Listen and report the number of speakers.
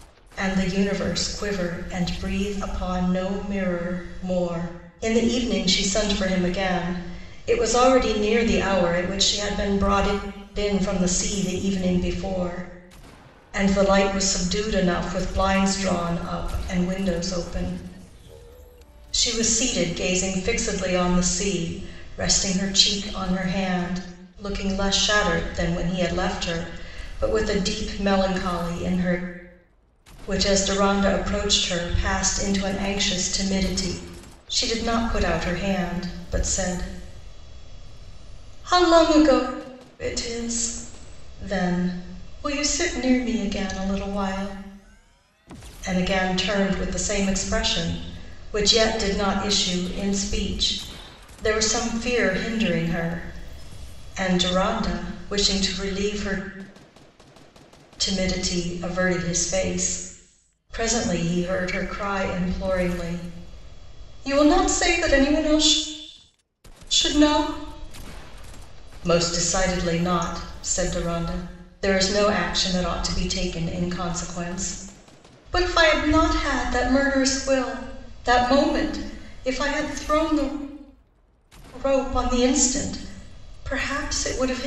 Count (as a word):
one